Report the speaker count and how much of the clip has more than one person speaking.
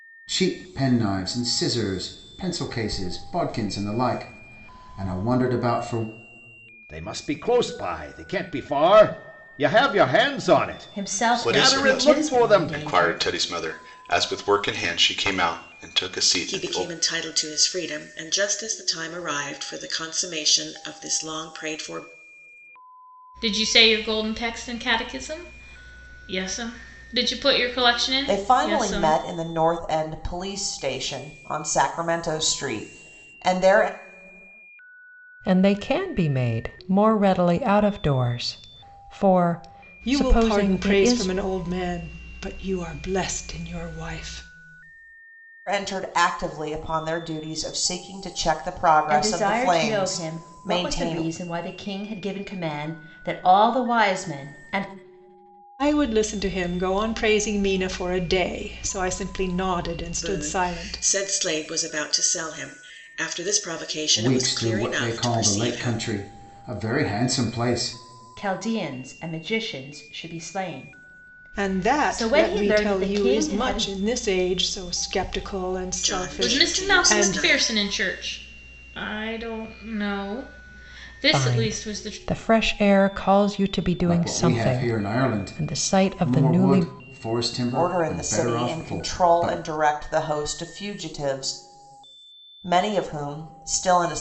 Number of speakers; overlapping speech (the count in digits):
9, about 21%